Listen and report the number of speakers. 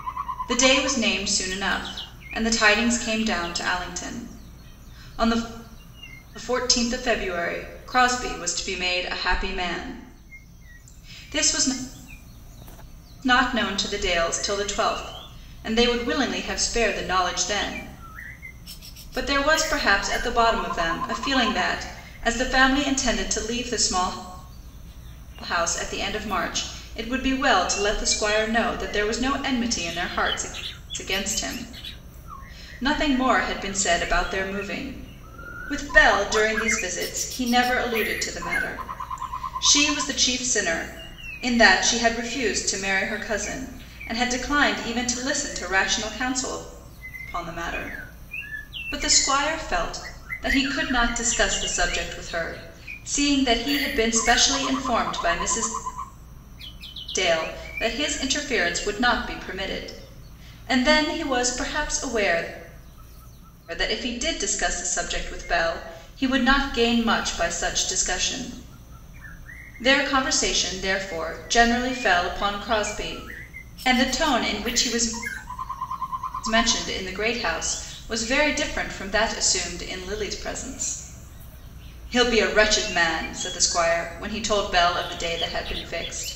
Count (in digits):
1